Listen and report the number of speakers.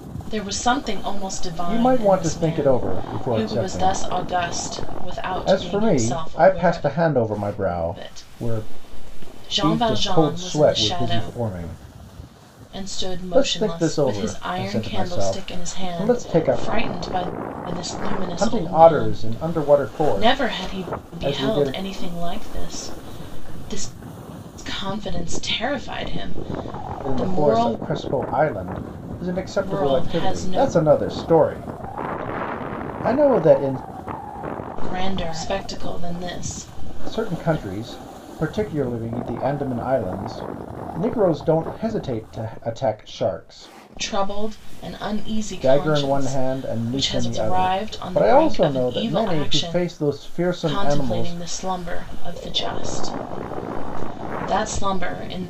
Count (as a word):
two